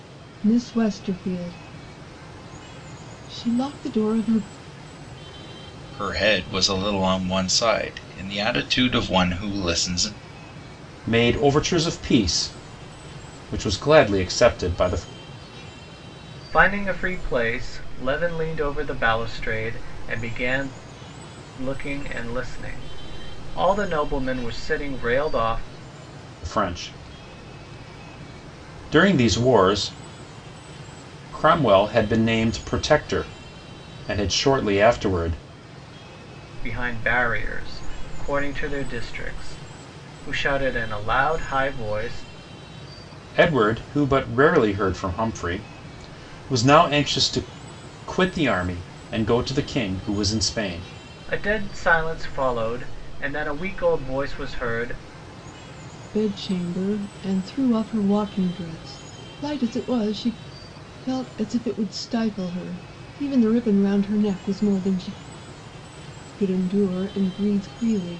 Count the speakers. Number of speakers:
4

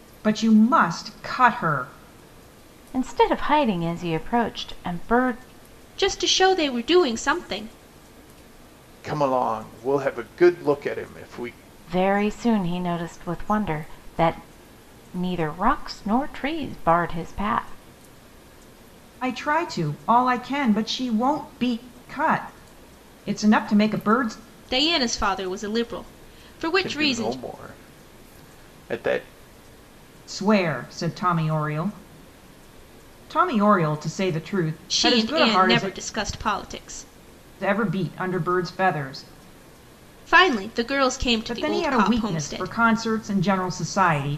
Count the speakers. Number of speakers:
4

